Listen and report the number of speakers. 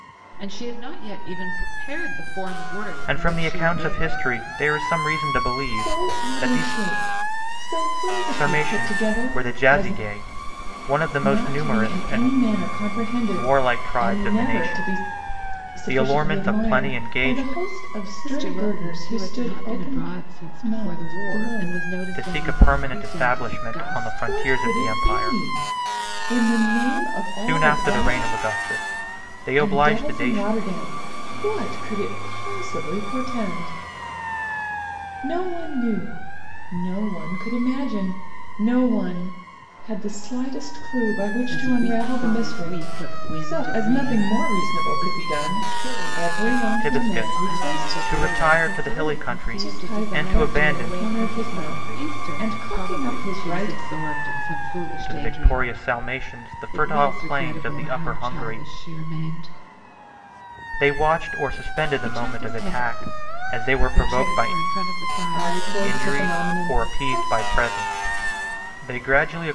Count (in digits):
3